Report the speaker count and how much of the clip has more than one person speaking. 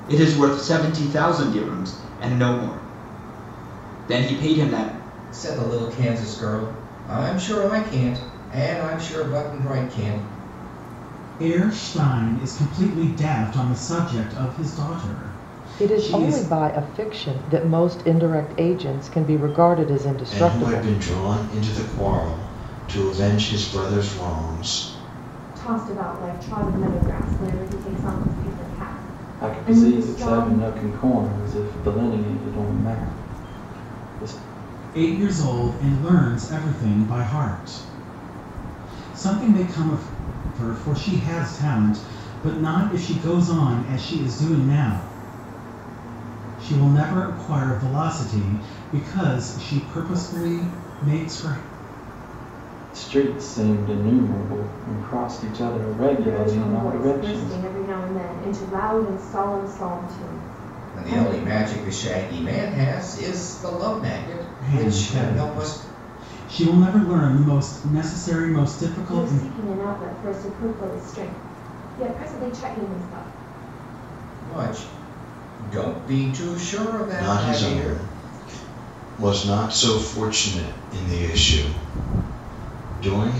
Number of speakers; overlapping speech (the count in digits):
7, about 8%